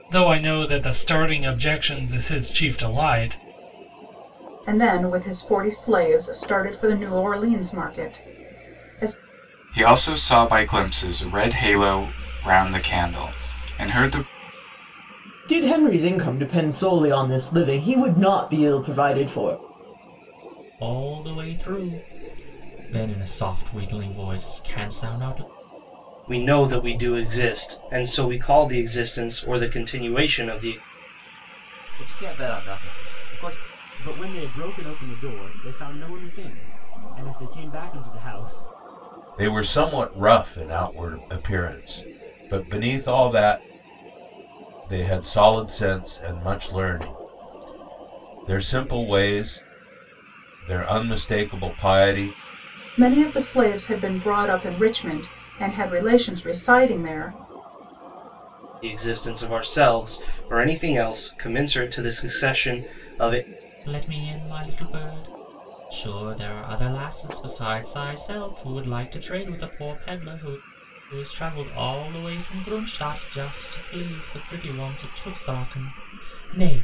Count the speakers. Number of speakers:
nine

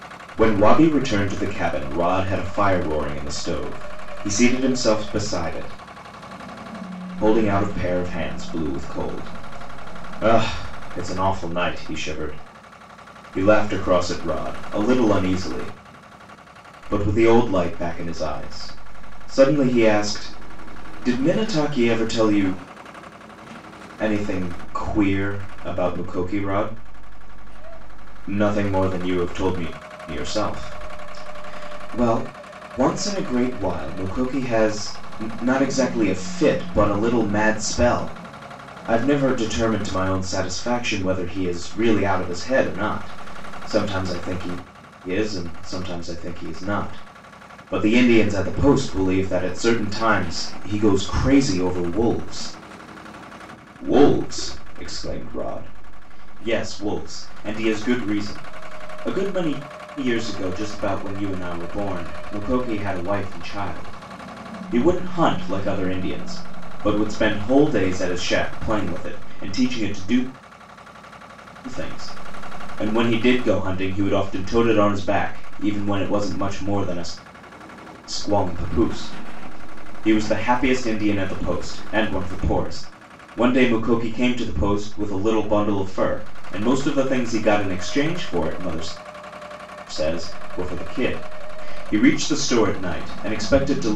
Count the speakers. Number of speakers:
one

